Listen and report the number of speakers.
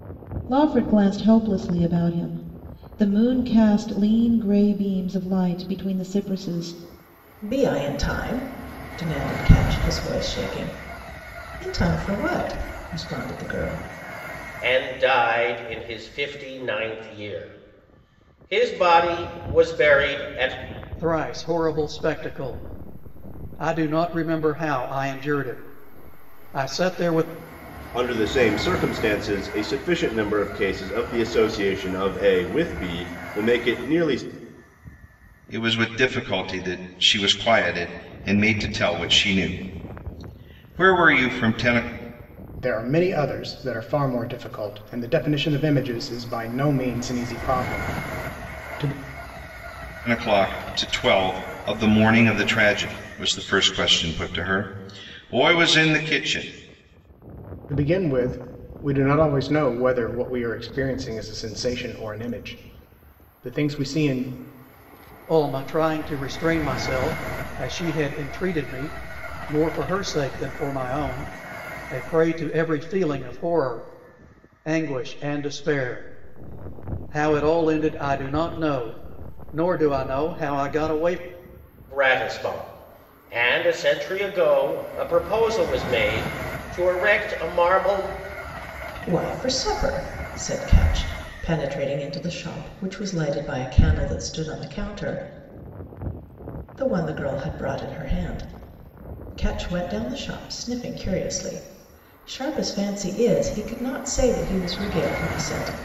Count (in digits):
7